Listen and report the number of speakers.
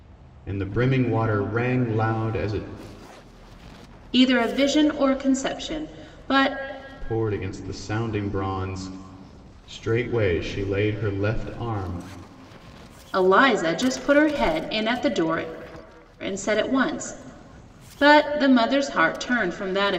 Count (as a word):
two